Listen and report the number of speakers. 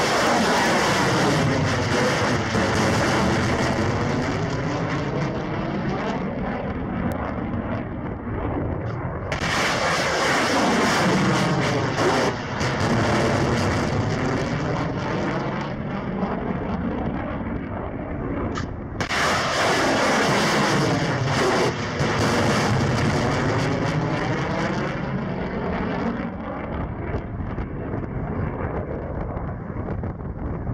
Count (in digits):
0